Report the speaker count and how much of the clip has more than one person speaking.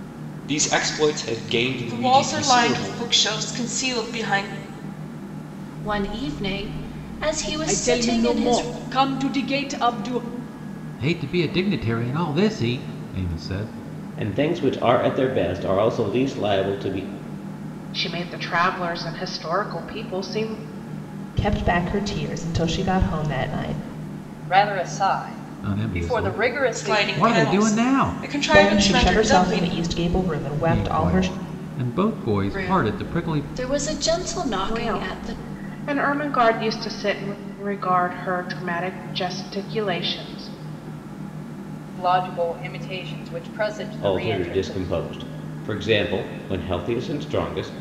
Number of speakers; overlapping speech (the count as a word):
nine, about 19%